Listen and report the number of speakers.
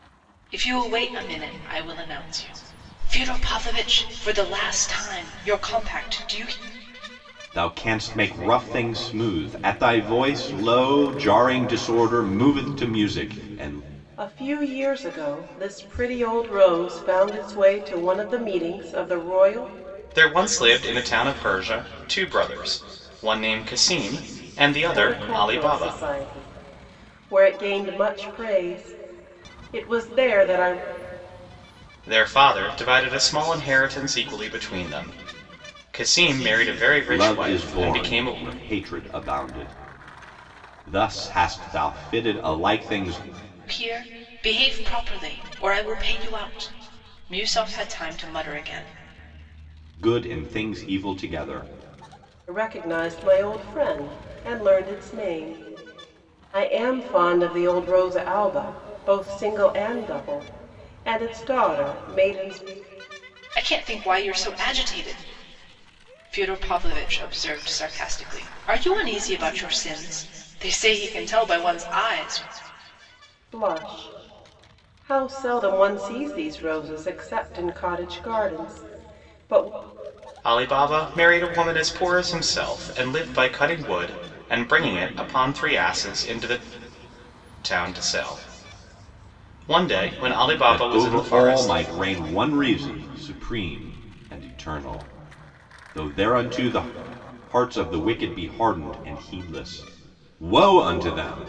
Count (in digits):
4